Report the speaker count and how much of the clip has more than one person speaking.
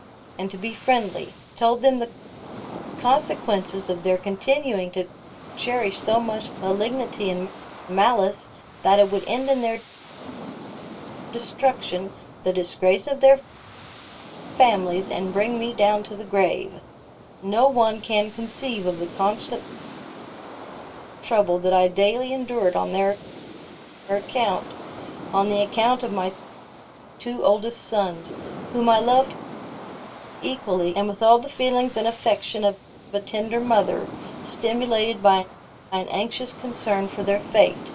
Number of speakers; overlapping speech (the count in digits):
1, no overlap